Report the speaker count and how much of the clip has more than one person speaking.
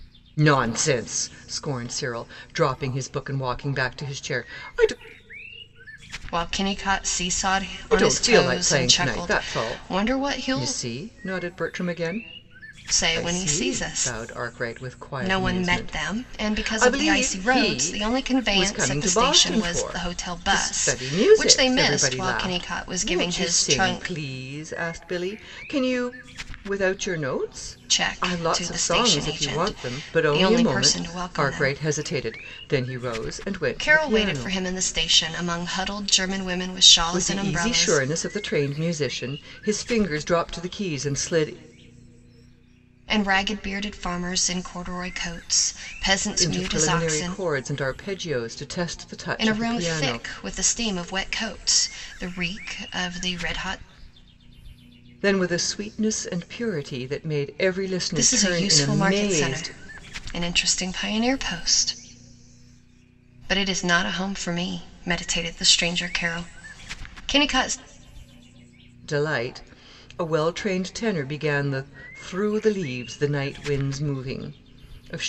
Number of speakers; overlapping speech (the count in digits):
2, about 29%